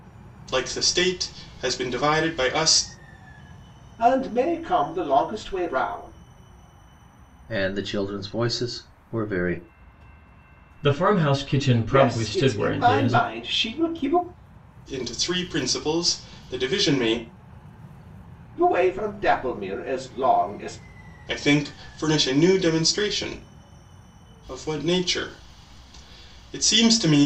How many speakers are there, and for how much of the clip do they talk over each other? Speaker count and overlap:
four, about 5%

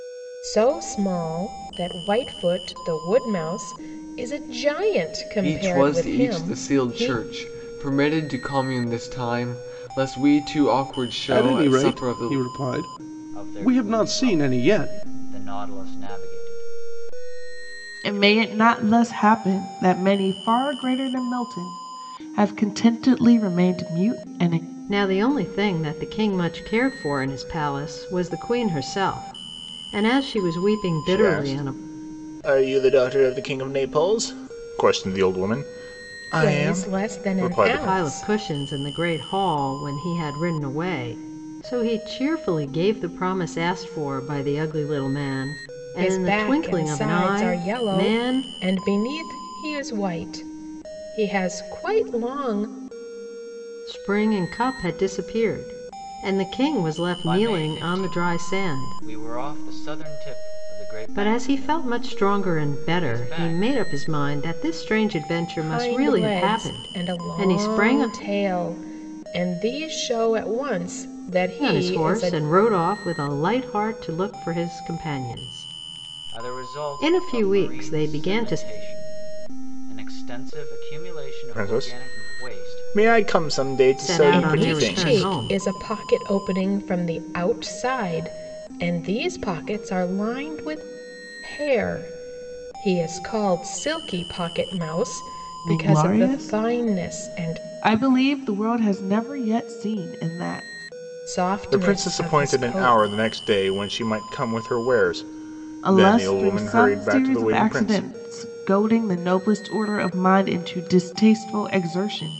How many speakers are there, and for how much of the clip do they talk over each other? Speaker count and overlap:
seven, about 26%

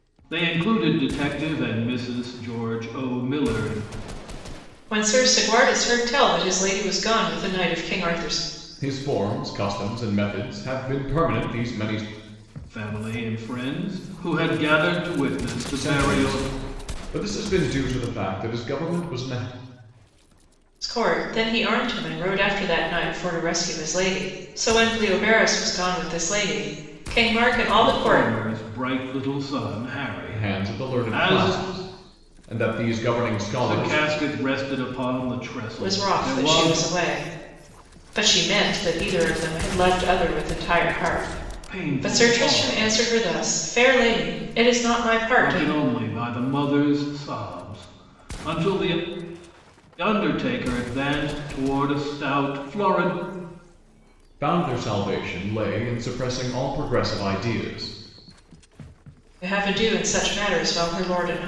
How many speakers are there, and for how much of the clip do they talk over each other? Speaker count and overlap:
three, about 9%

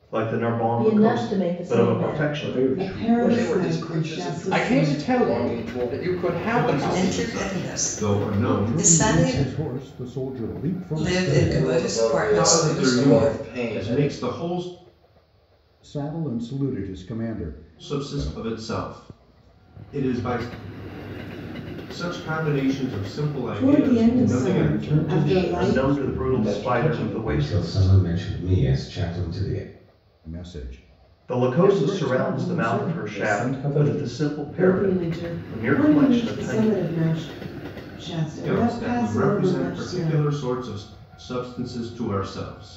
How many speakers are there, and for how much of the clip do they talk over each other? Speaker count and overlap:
ten, about 58%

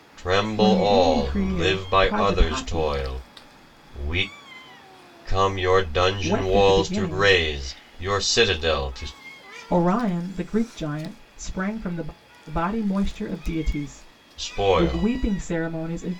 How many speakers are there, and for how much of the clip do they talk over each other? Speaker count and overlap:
two, about 26%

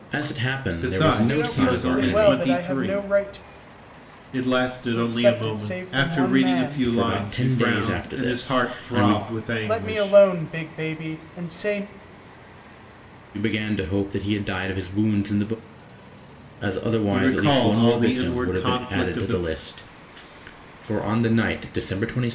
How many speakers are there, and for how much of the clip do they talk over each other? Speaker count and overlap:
three, about 43%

